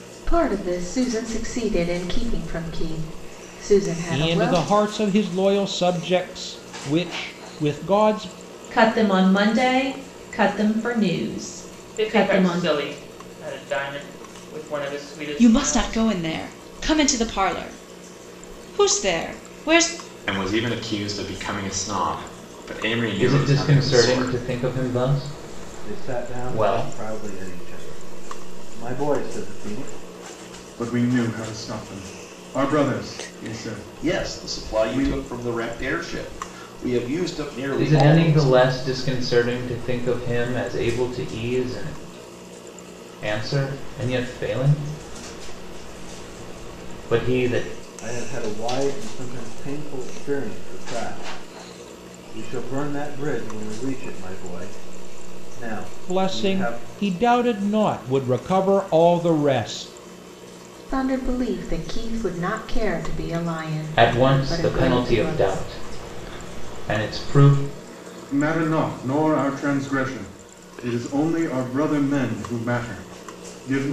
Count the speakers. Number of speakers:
10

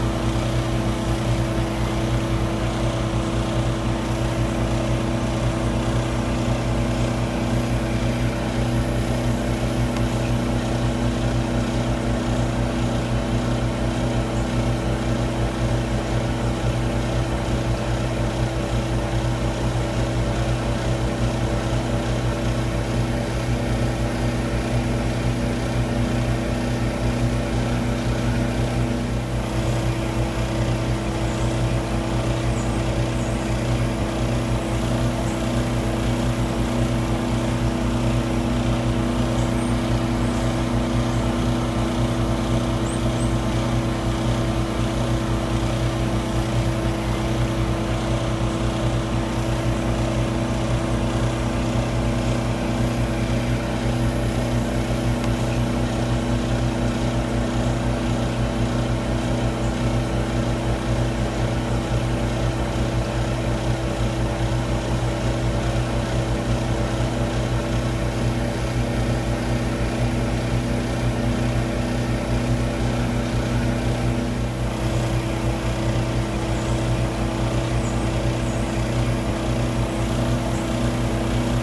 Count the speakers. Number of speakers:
0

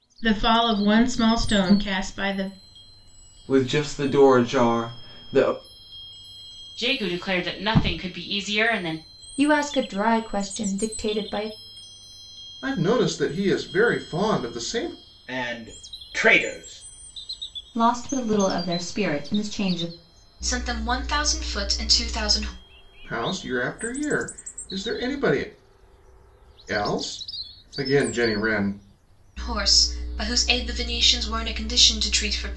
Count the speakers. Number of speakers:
8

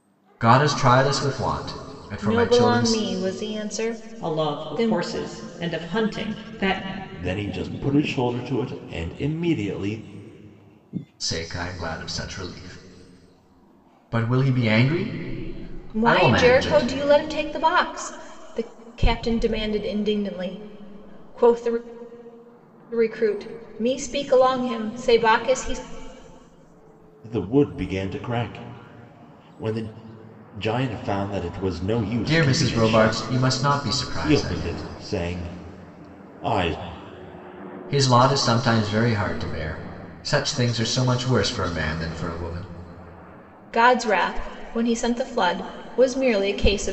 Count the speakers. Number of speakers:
4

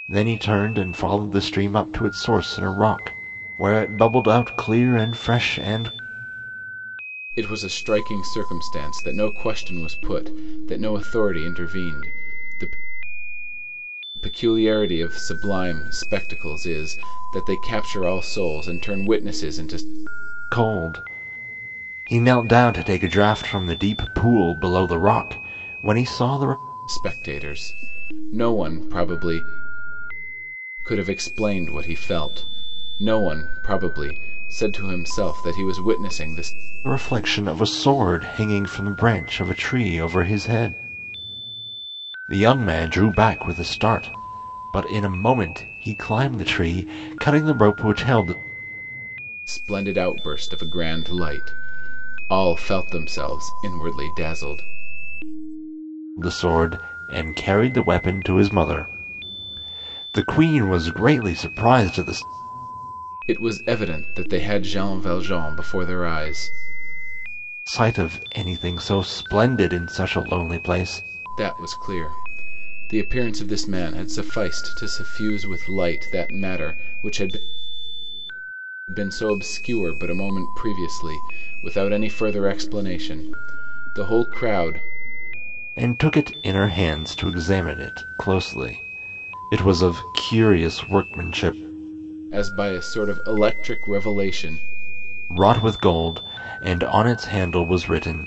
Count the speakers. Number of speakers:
2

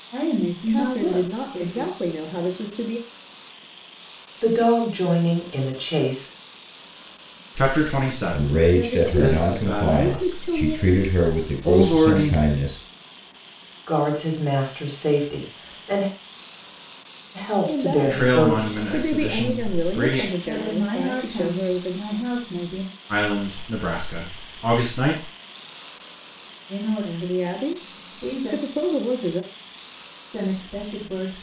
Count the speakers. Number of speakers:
5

